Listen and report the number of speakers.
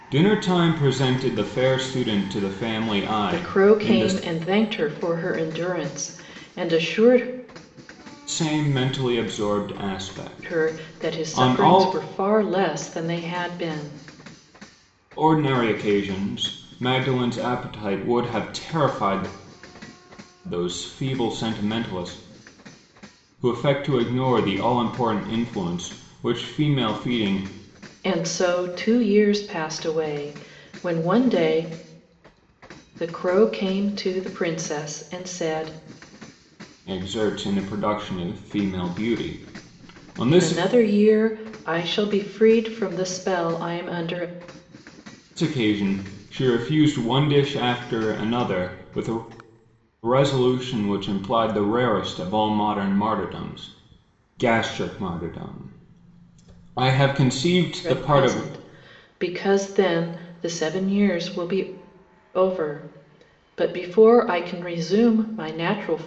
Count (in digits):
2